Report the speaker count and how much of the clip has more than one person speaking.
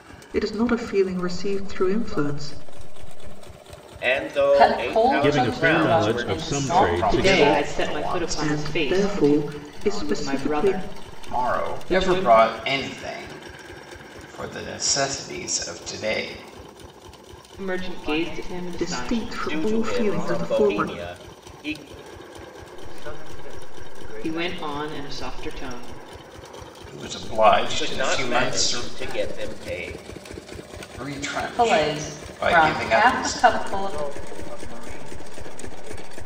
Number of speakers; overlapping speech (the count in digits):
7, about 47%